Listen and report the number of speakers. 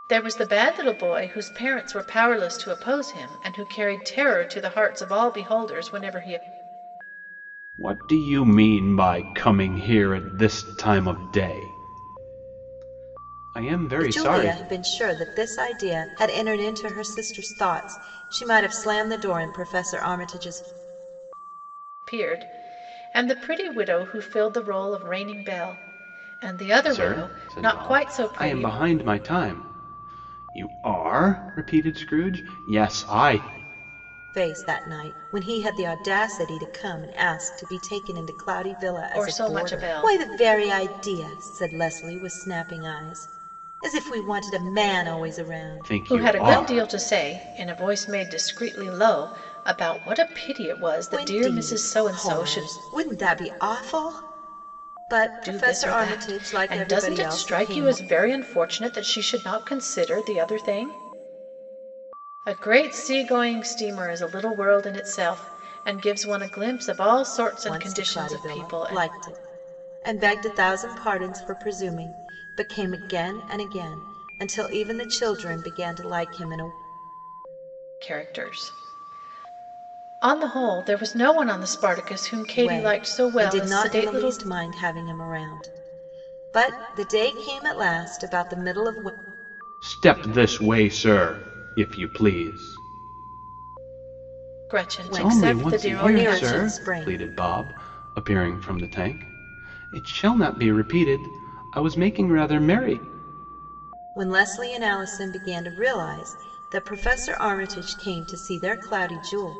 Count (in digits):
3